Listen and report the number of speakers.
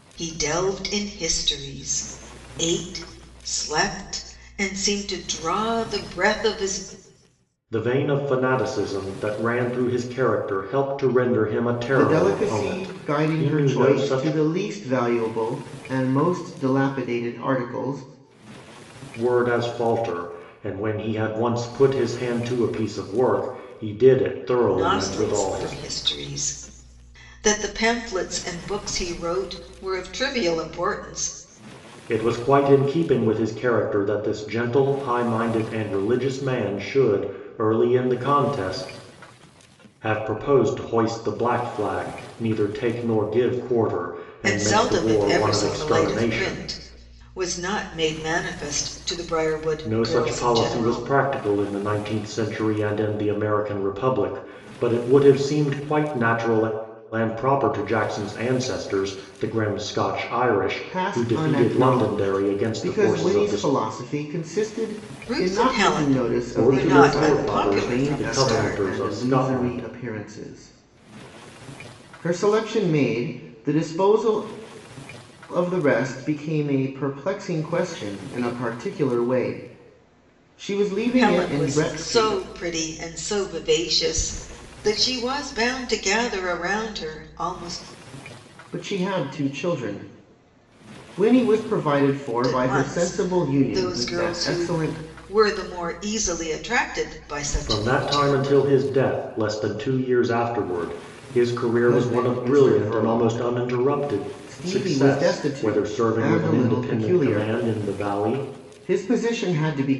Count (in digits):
3